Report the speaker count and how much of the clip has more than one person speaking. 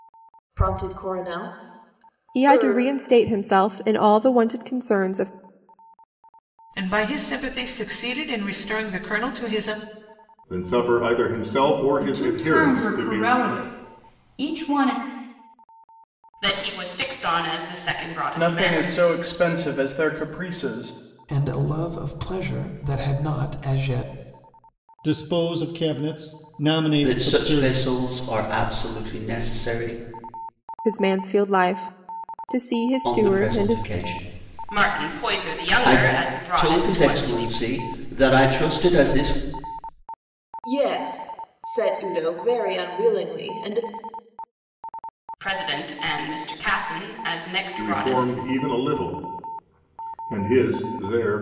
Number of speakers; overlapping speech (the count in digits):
10, about 14%